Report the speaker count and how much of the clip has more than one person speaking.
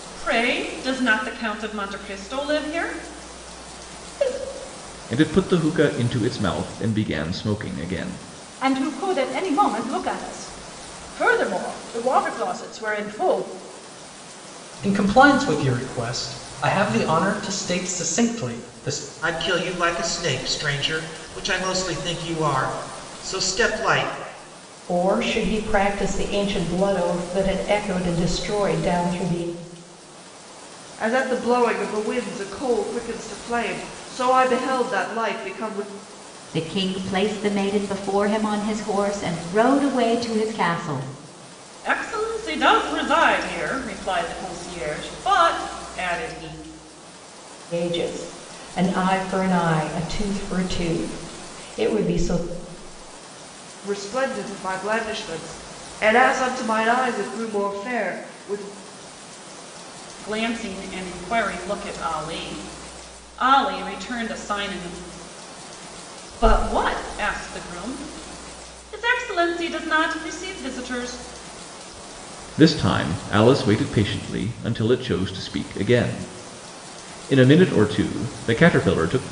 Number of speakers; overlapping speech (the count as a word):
eight, no overlap